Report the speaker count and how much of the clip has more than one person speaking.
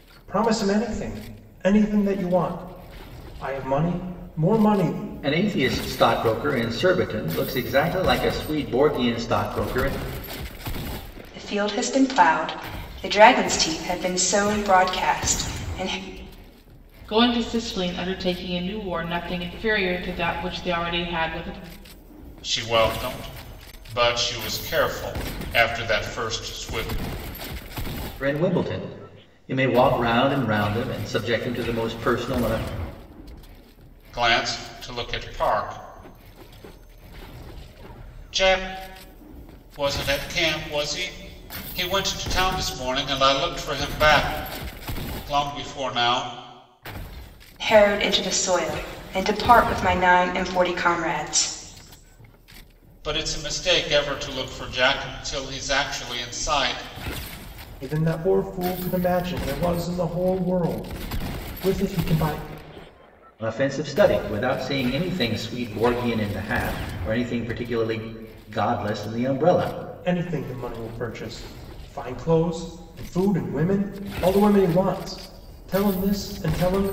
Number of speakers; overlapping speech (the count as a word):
five, no overlap